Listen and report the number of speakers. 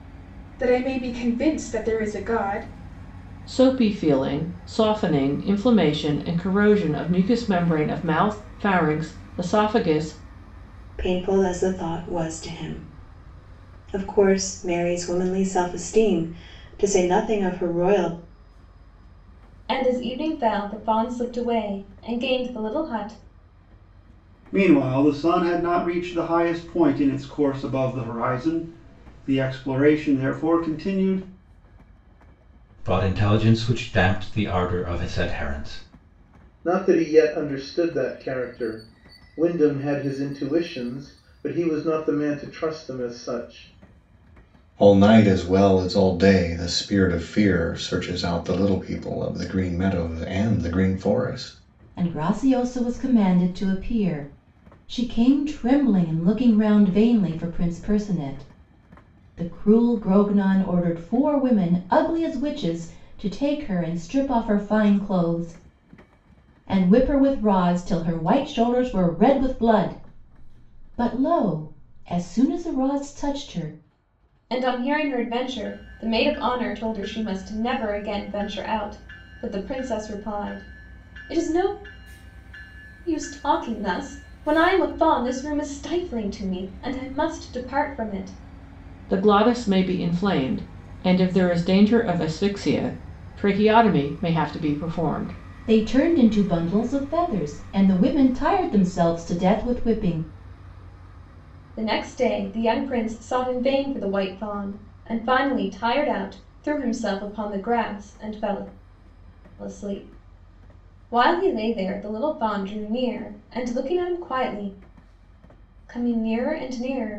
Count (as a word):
nine